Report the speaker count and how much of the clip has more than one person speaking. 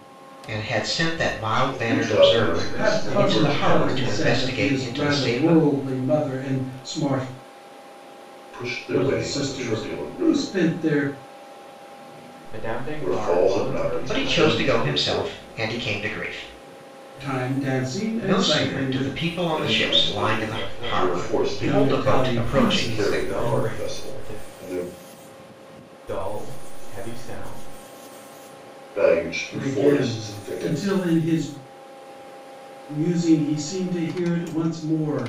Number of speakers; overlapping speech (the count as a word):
four, about 44%